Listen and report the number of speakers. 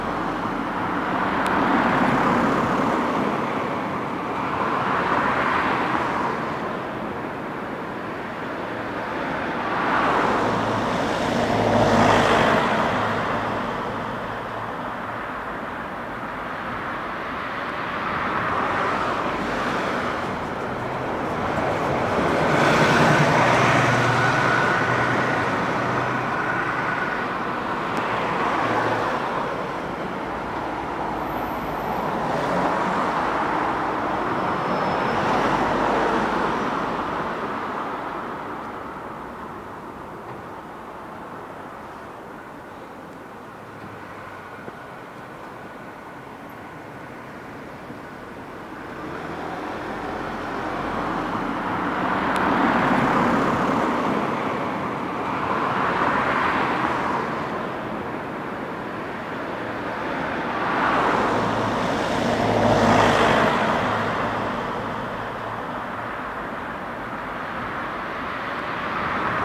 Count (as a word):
zero